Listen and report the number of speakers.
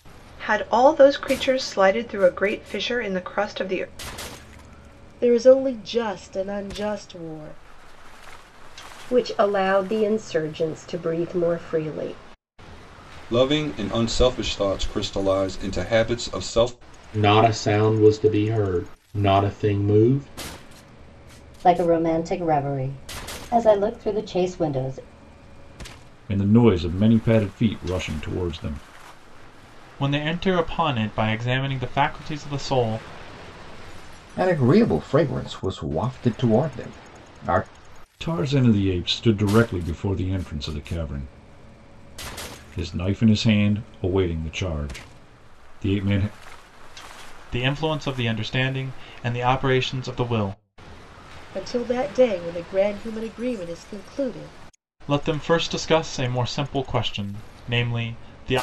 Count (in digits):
9